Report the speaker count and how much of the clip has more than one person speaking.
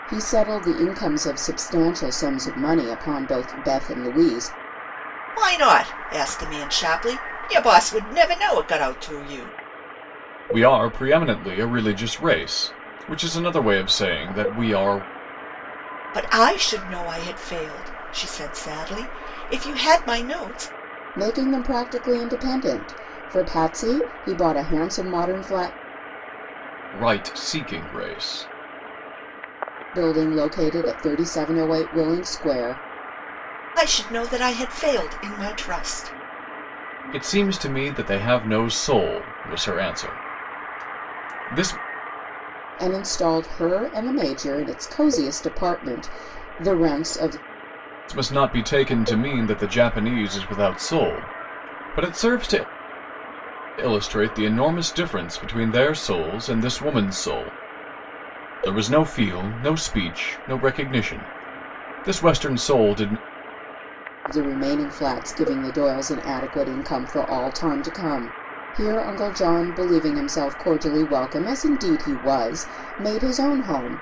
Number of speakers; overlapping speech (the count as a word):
three, no overlap